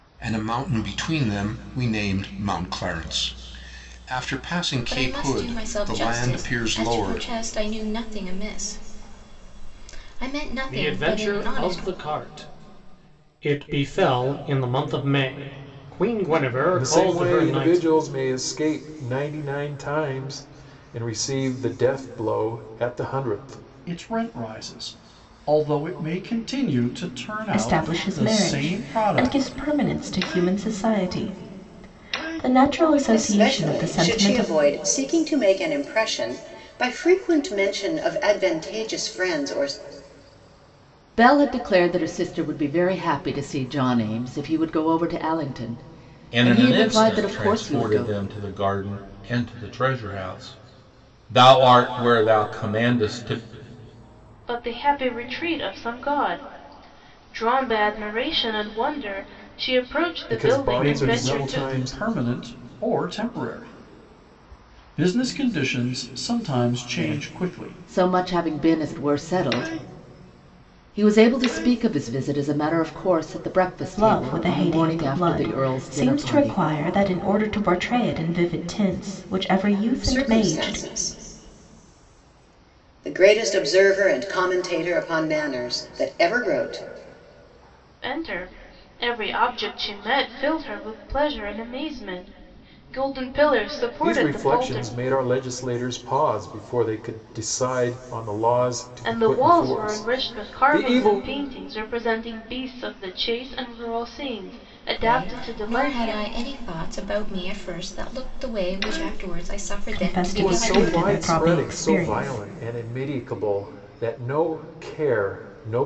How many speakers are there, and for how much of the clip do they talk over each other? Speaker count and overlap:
ten, about 20%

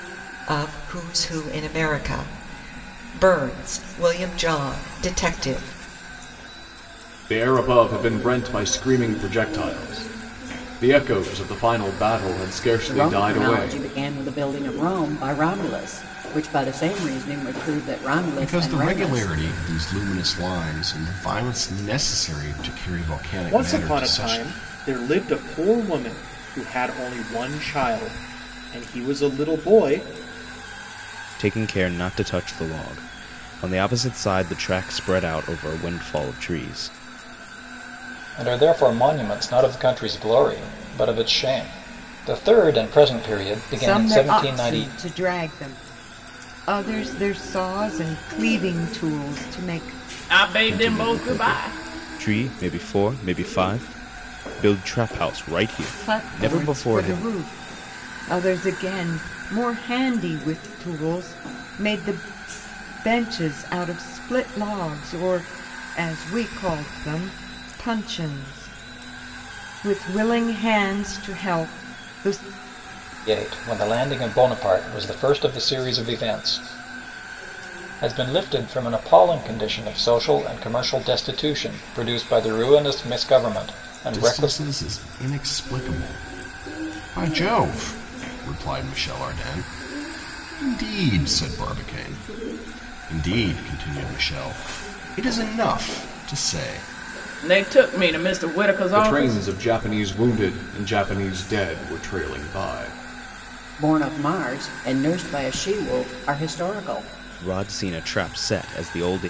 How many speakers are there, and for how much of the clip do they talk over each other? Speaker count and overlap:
nine, about 7%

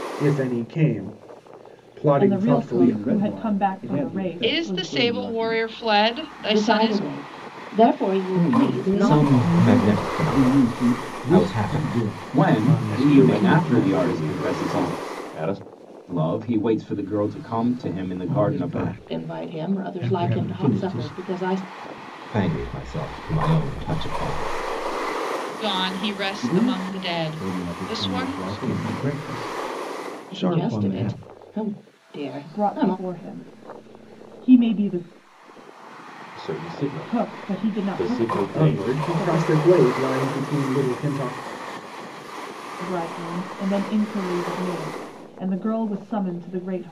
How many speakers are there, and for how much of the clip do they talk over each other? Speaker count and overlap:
ten, about 41%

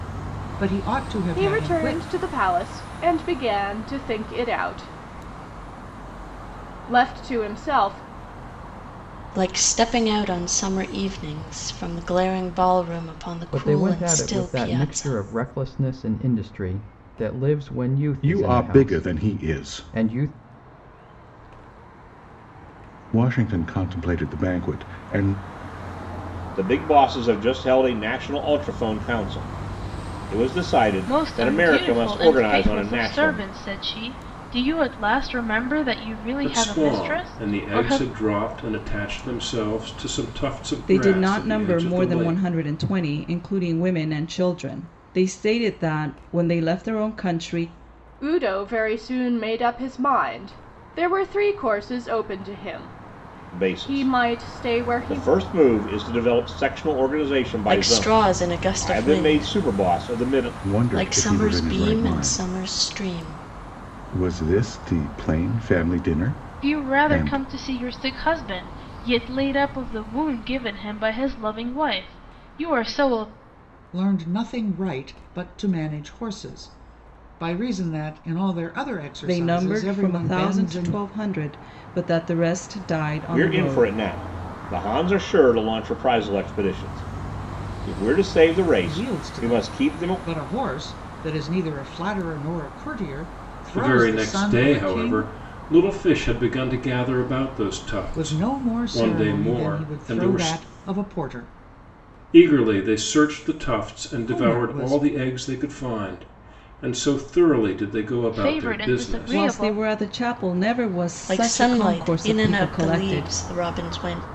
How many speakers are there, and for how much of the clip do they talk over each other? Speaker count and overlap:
nine, about 29%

